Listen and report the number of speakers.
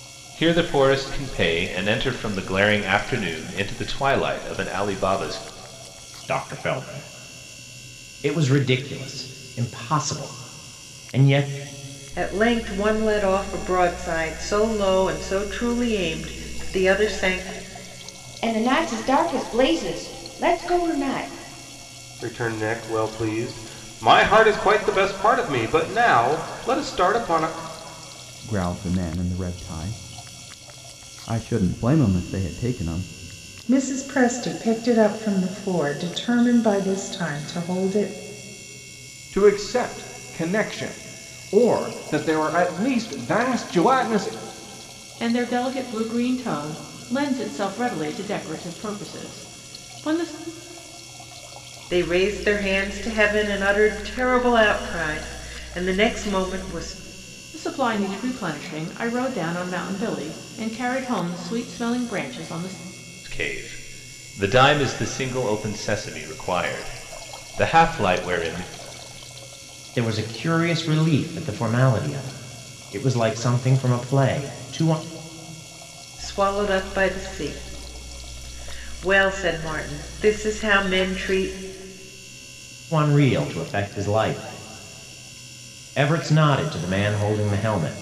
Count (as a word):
nine